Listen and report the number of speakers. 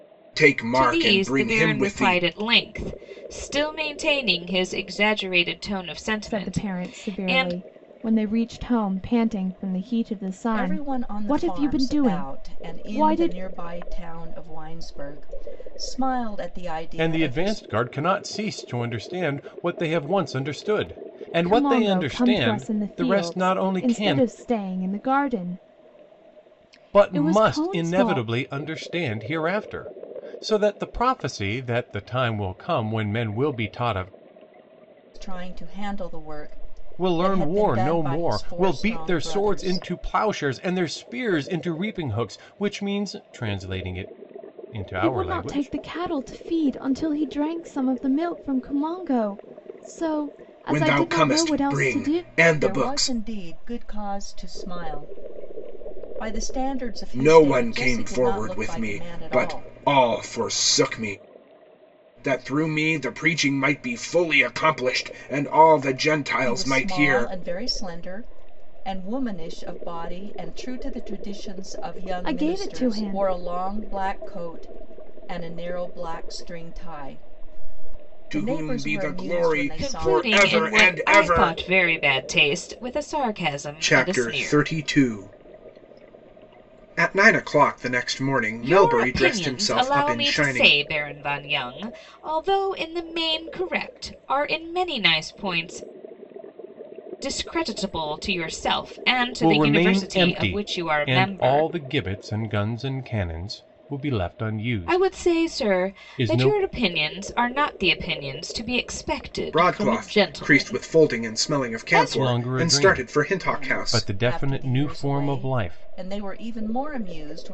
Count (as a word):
five